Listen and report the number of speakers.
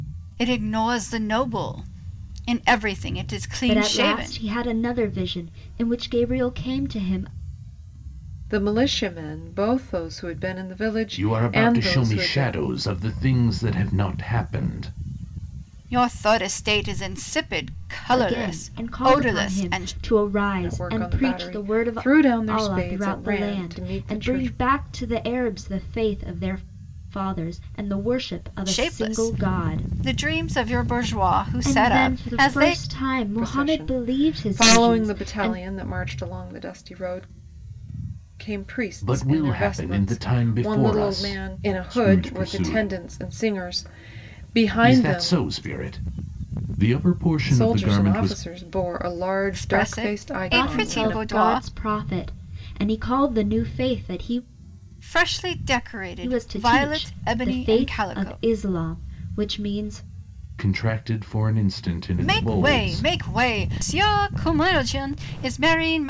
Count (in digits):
4